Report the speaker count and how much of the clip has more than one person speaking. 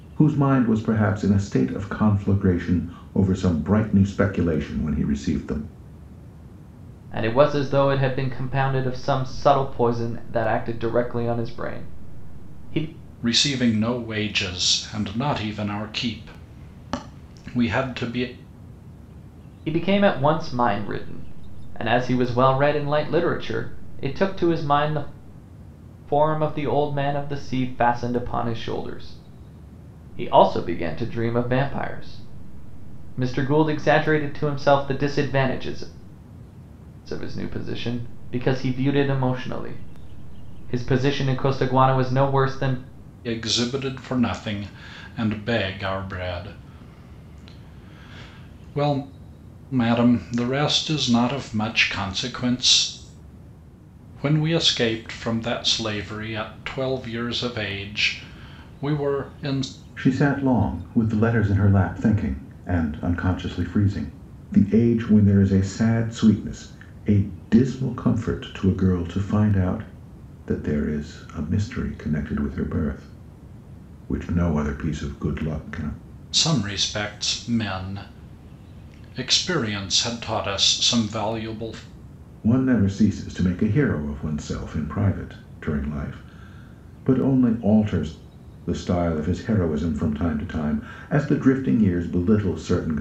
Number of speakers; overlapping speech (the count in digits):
3, no overlap